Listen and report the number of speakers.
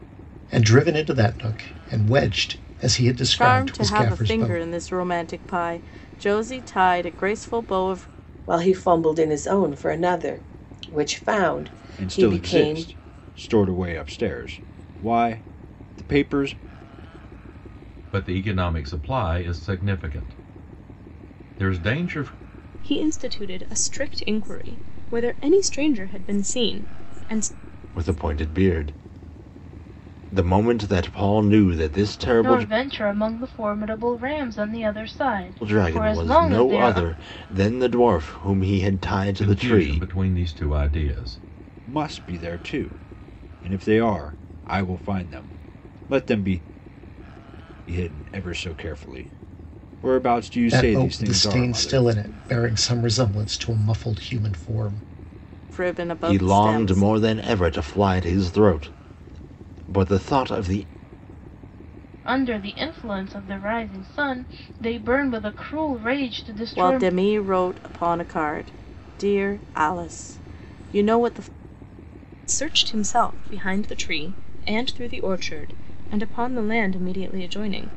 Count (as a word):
eight